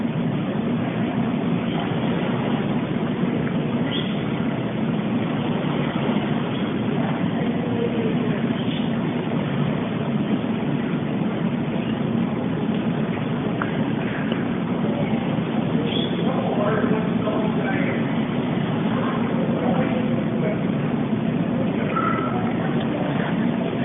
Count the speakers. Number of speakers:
0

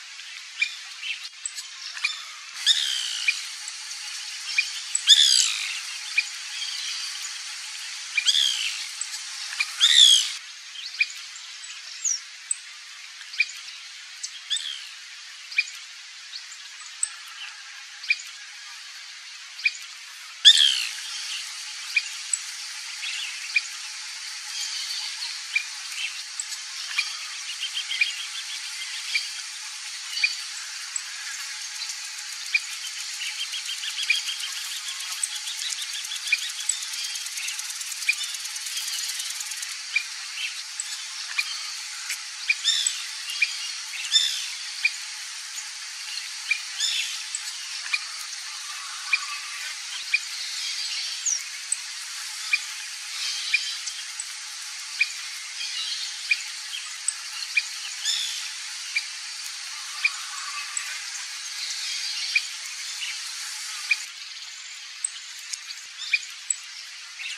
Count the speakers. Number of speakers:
0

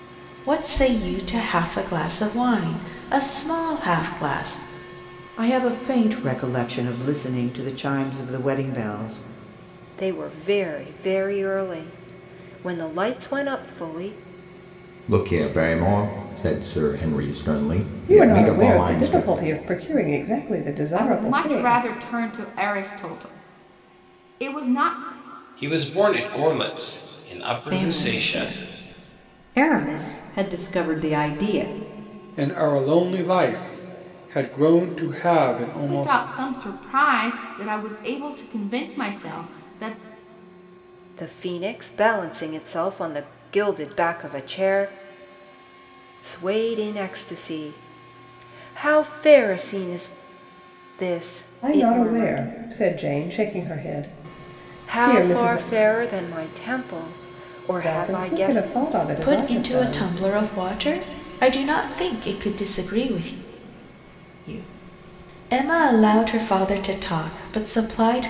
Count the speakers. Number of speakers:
9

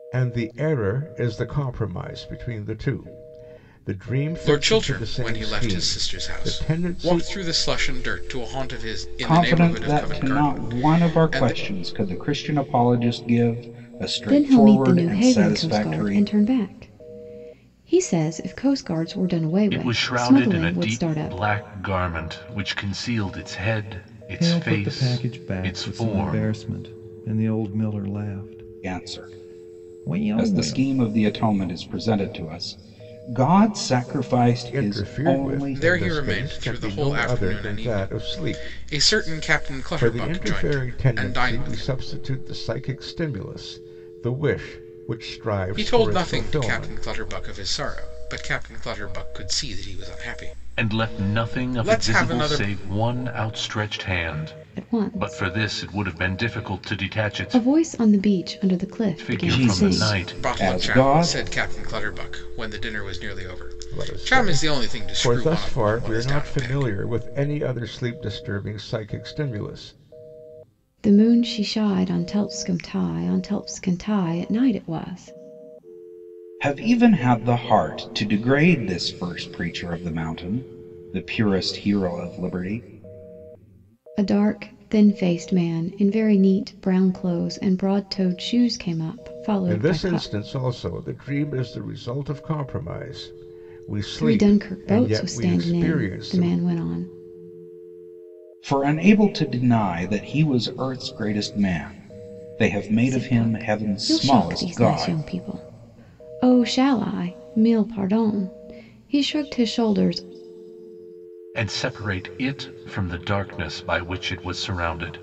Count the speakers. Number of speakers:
6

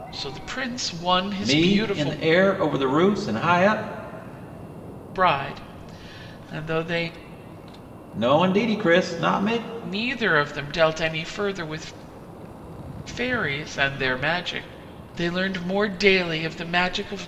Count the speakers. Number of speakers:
2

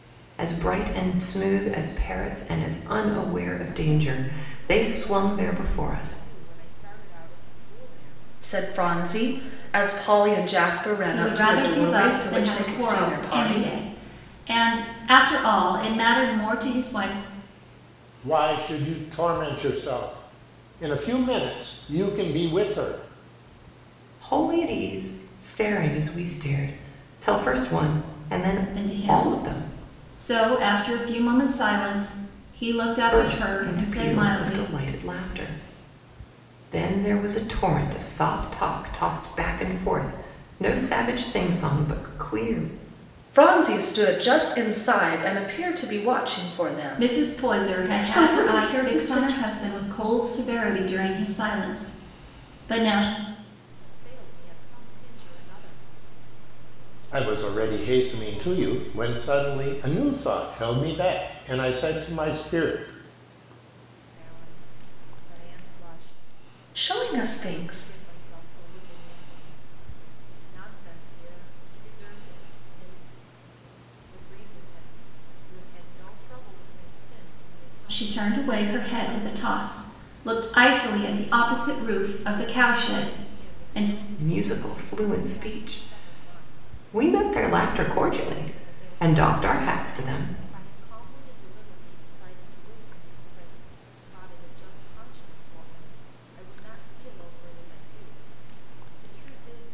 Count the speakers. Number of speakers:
5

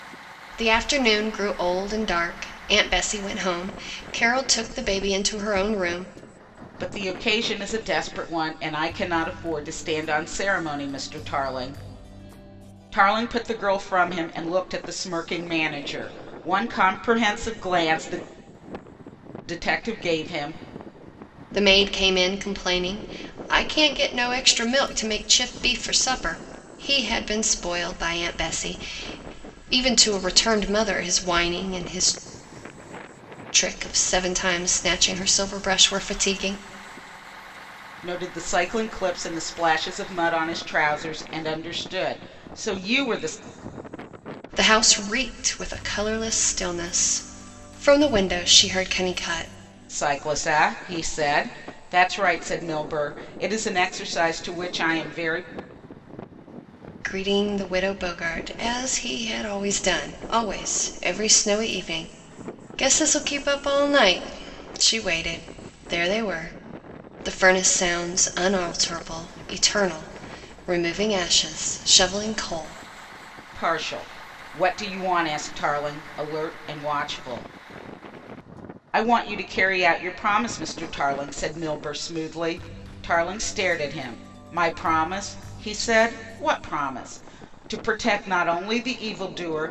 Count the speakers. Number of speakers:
2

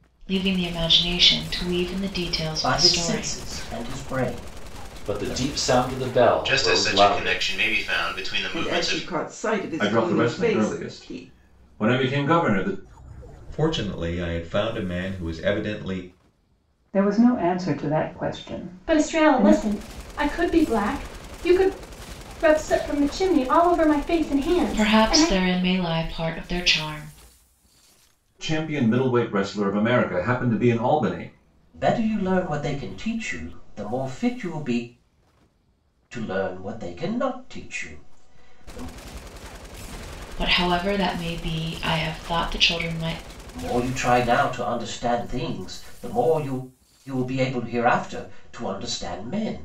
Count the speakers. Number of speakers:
9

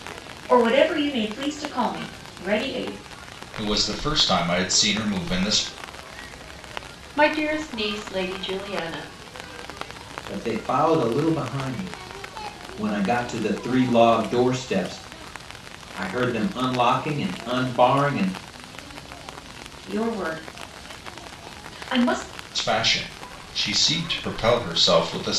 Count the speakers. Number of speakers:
4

